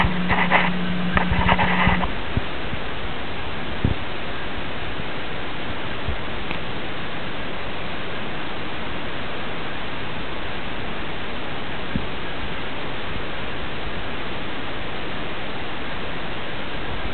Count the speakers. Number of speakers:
0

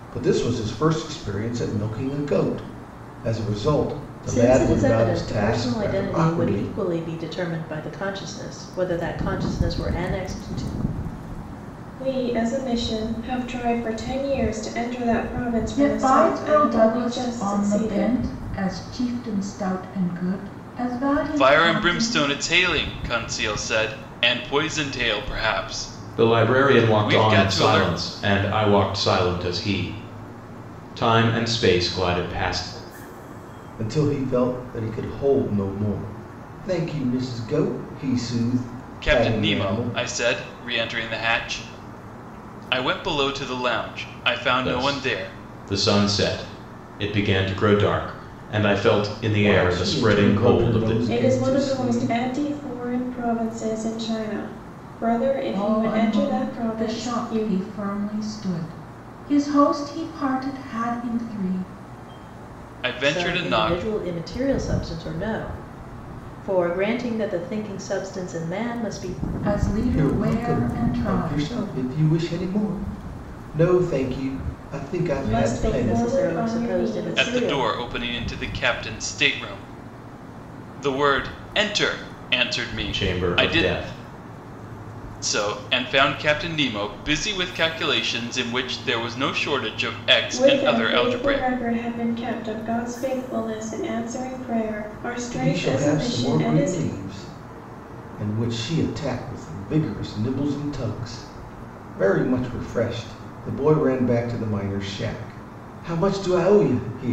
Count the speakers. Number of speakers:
6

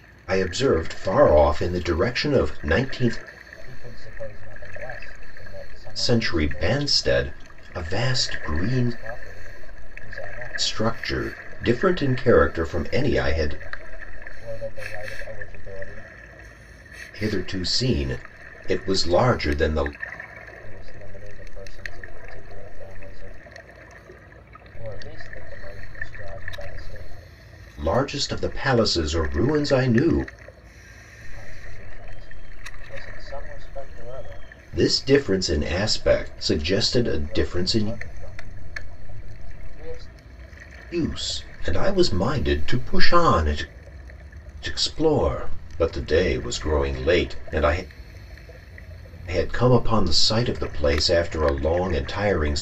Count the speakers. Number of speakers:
2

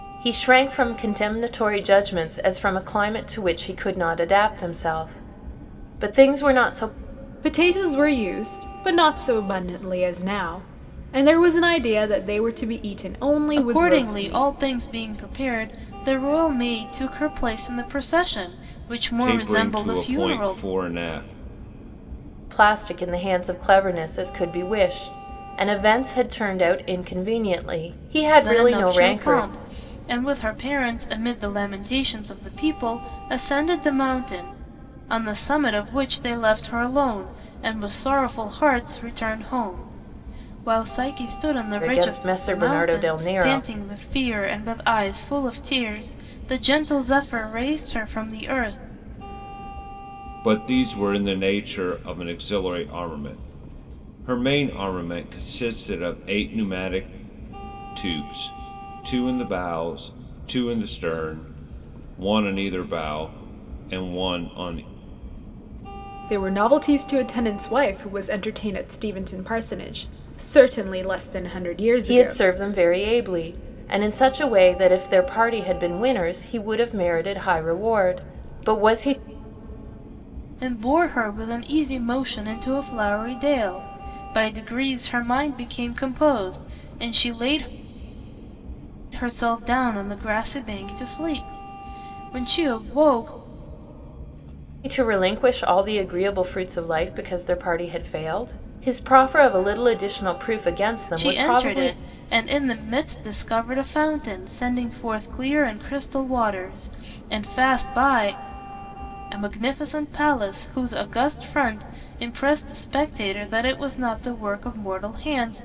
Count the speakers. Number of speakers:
4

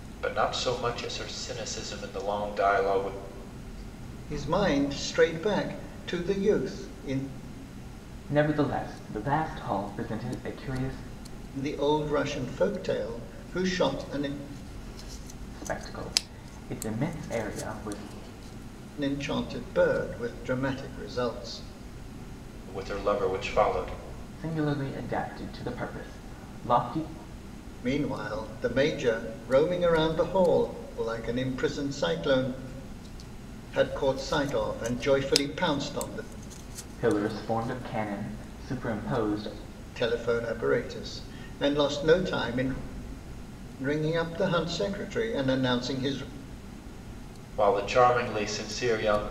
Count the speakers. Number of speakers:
3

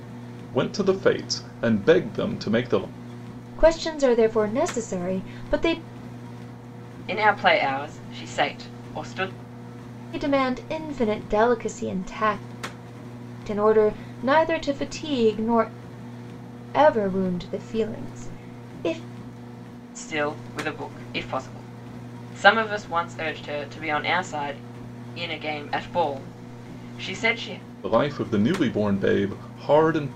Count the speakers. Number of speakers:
3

